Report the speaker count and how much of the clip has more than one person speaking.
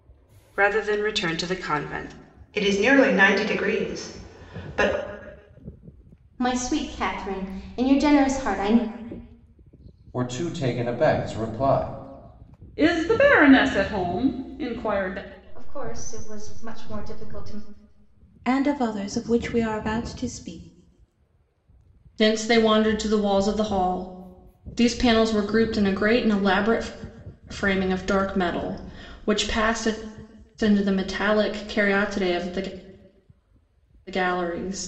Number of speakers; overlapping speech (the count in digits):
8, no overlap